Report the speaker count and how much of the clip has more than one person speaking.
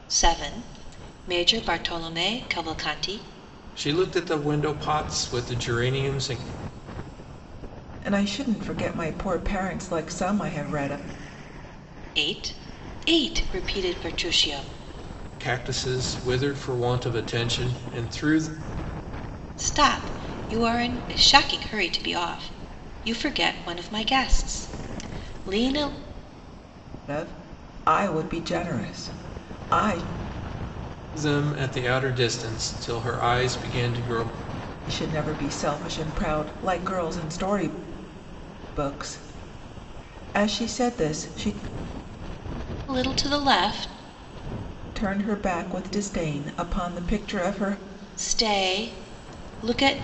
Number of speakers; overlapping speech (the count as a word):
three, no overlap